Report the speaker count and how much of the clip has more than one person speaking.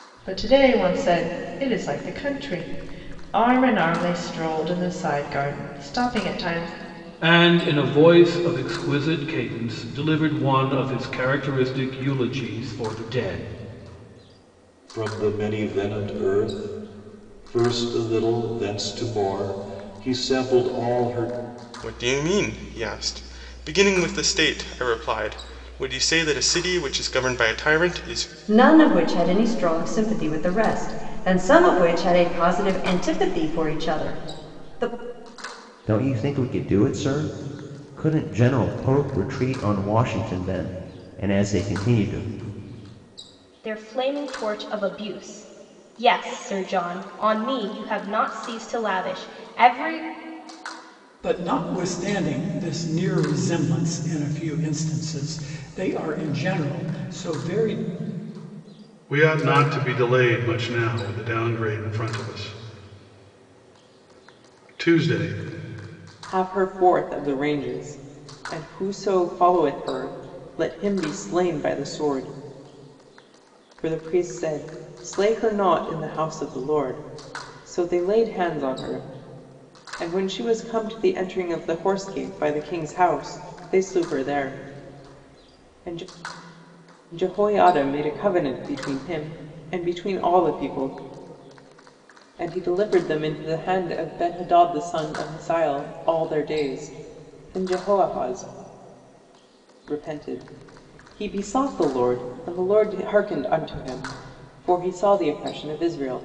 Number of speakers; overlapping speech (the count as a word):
ten, no overlap